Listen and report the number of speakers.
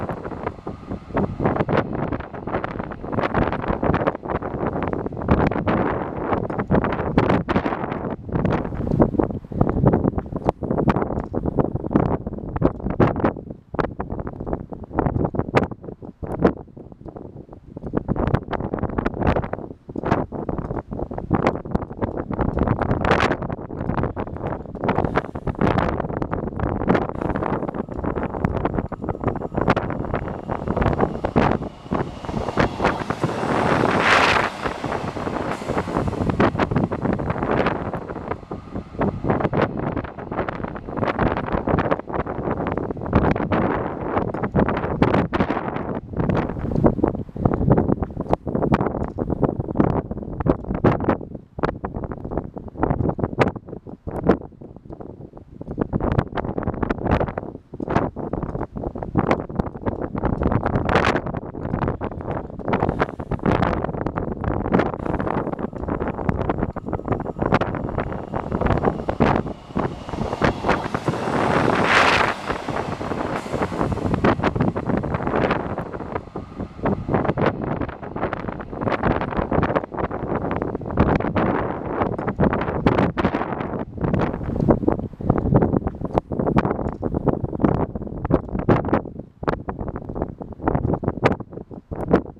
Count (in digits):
0